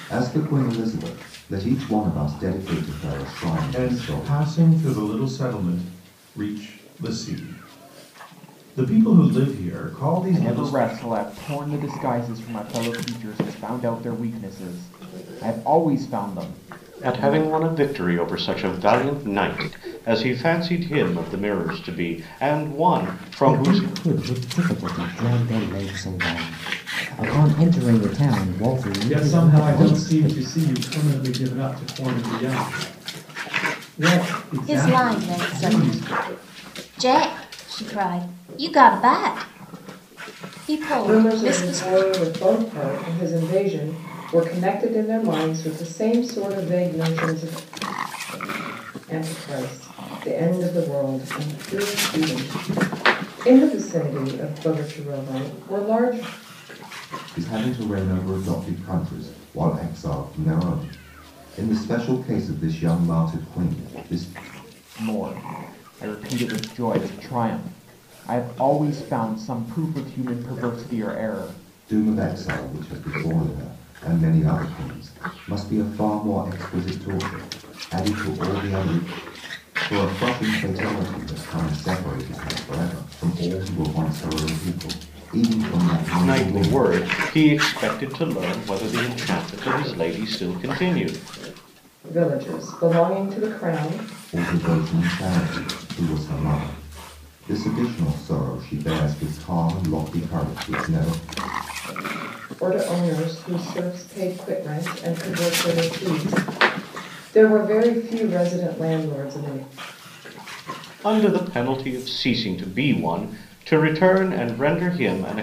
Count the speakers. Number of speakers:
8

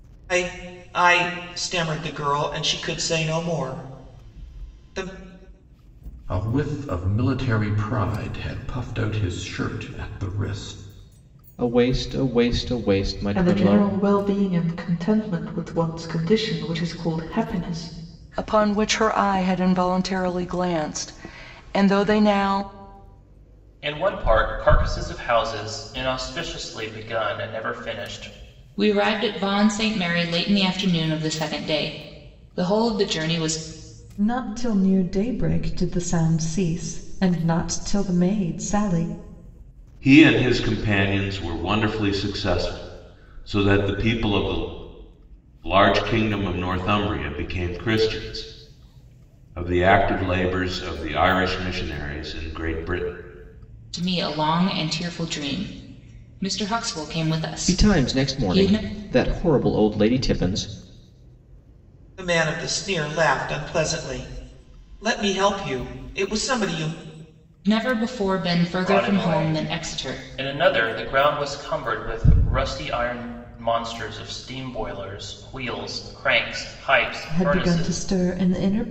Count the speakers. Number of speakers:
9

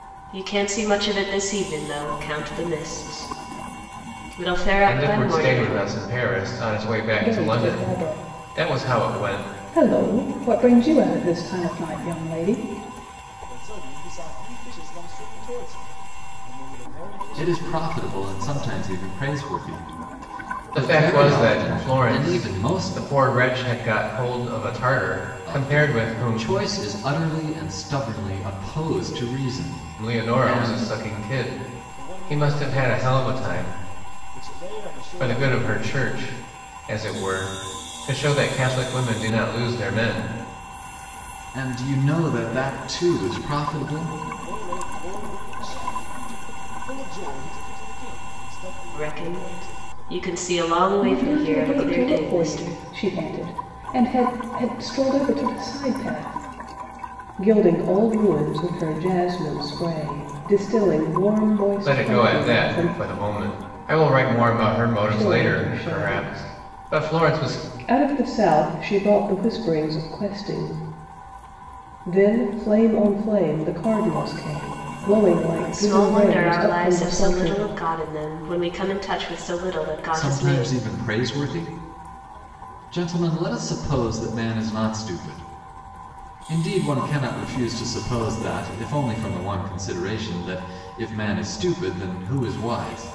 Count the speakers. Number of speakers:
5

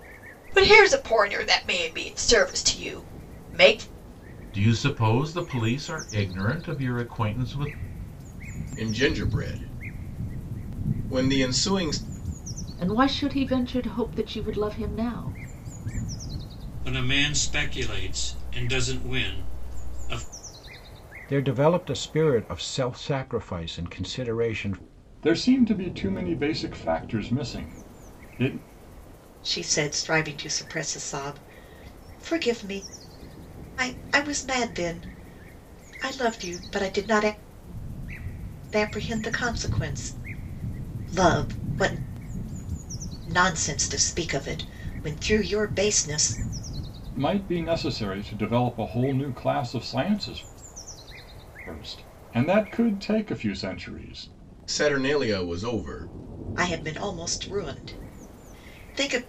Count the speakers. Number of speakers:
8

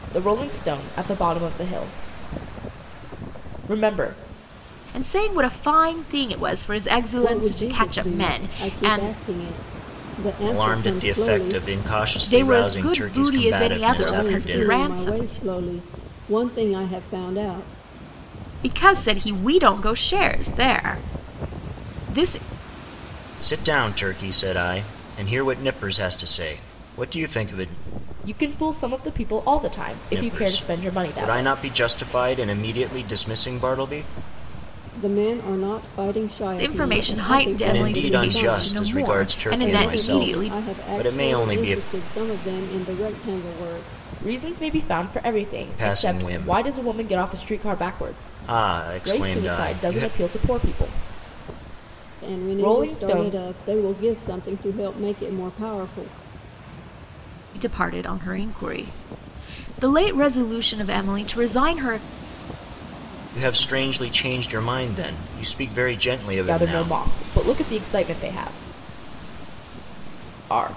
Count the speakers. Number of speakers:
4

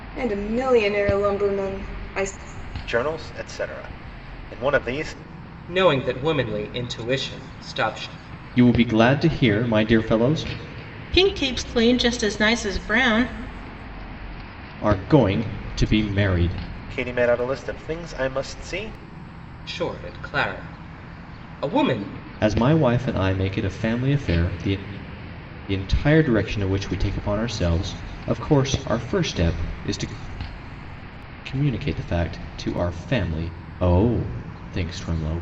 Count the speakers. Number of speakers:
5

